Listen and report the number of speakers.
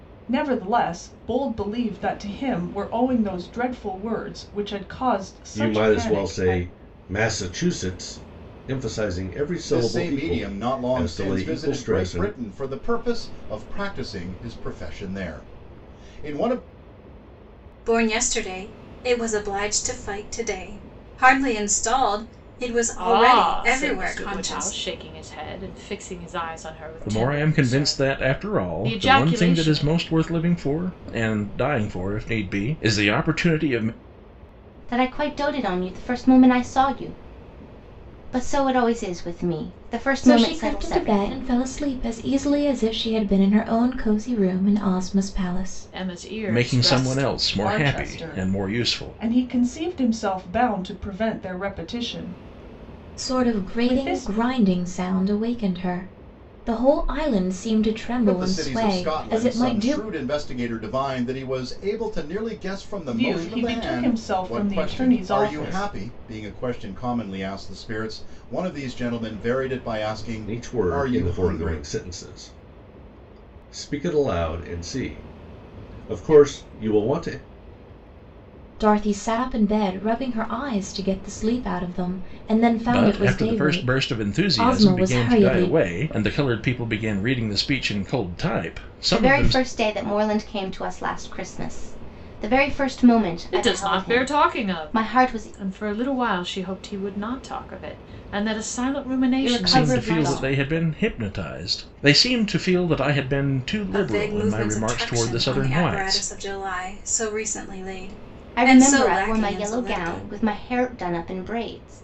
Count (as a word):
eight